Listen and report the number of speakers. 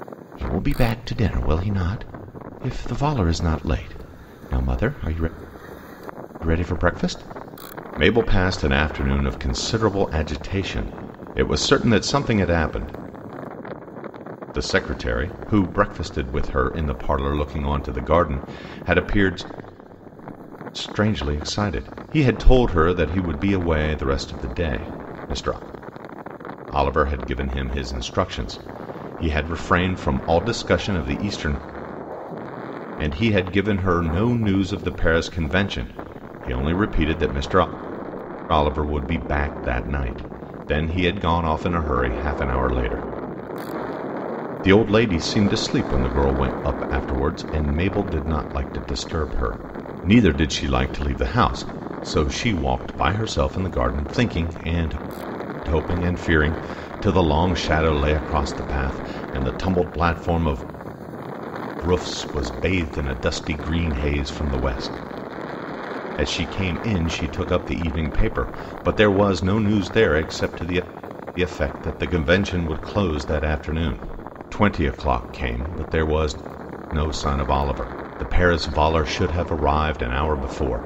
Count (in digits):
1